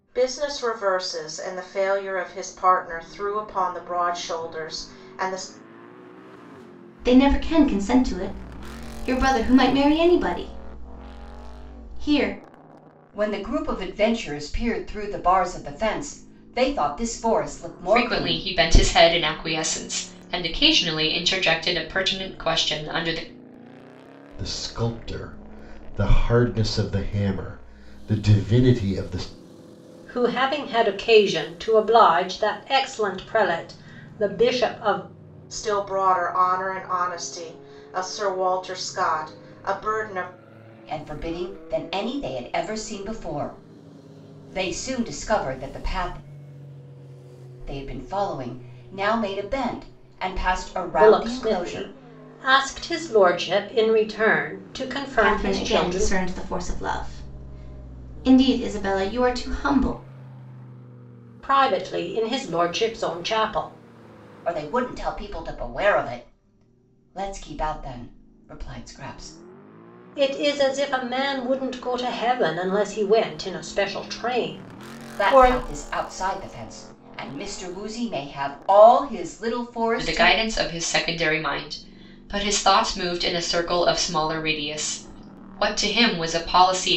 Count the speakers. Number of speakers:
6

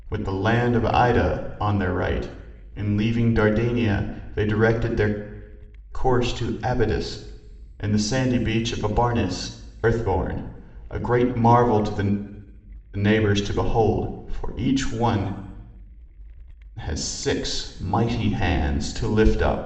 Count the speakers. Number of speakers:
1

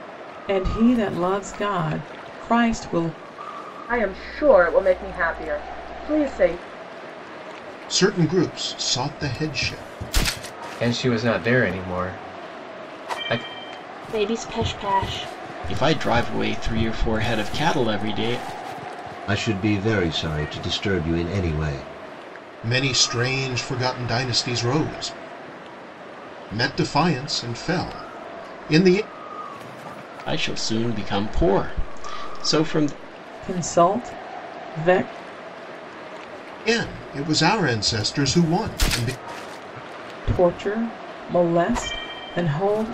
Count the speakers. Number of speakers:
7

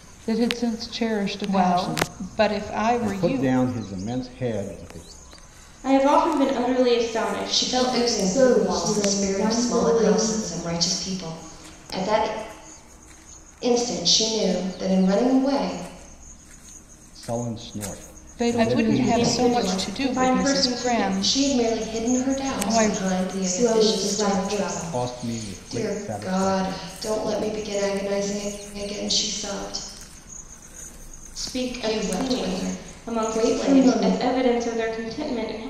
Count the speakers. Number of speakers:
6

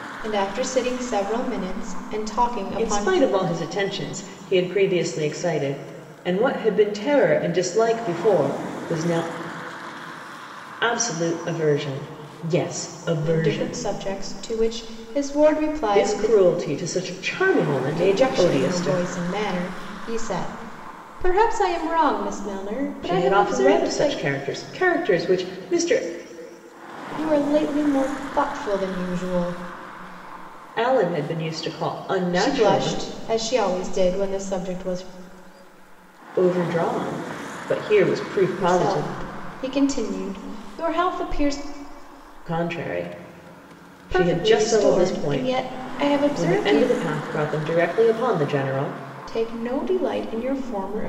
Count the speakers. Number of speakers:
2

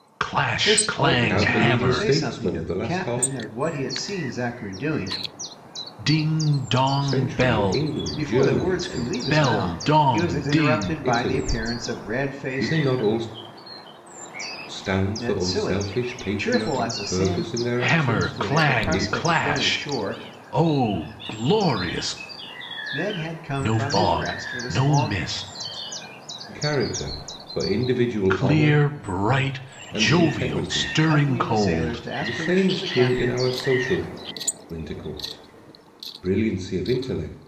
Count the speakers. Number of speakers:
3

